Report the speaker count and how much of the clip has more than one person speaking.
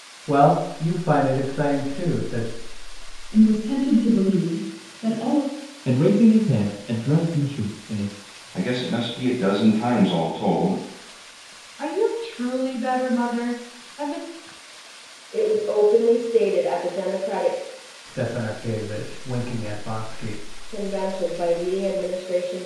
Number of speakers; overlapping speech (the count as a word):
six, no overlap